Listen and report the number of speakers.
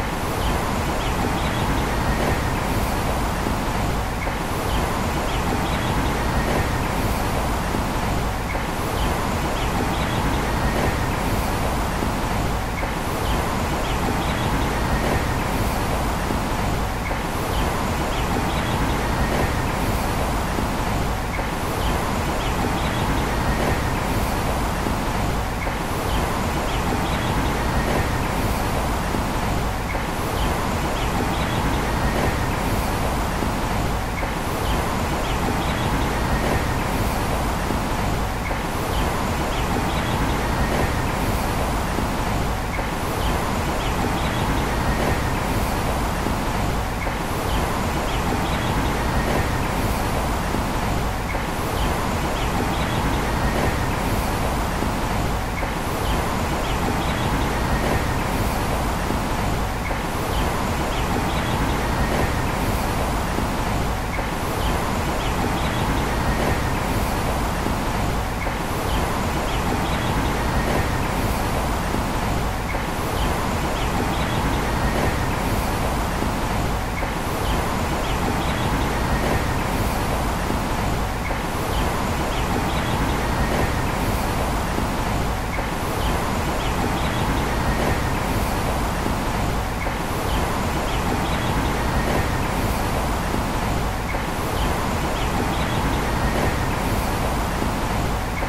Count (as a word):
zero